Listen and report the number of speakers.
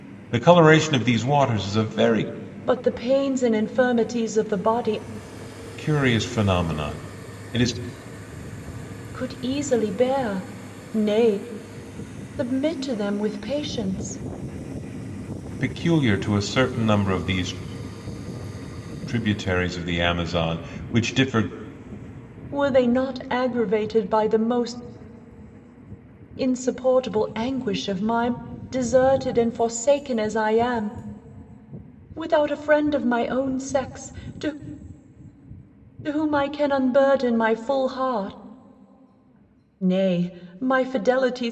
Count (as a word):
two